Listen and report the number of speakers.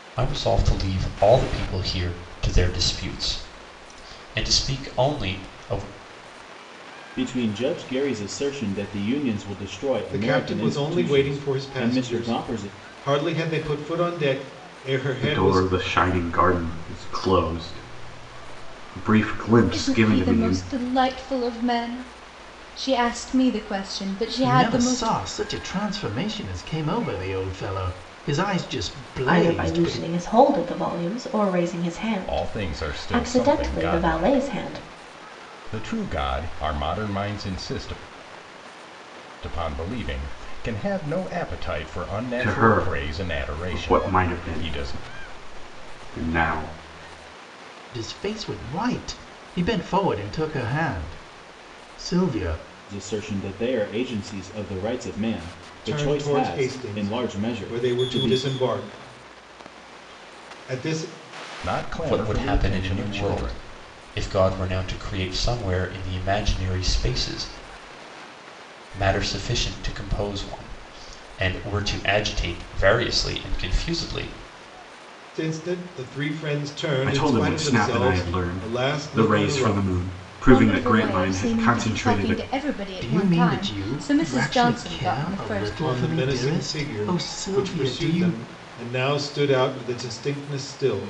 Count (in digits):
8